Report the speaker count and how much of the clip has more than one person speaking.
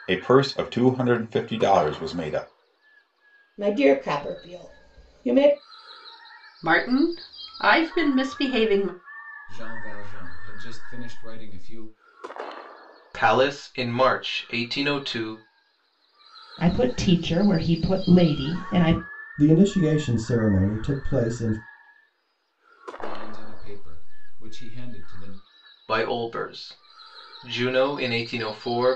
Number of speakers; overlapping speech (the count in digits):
7, no overlap